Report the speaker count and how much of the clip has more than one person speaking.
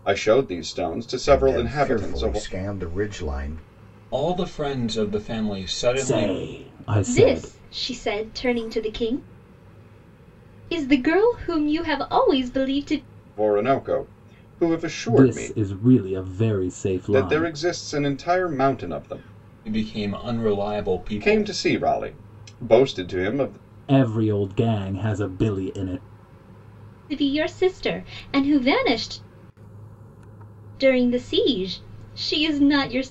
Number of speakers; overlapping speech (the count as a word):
five, about 10%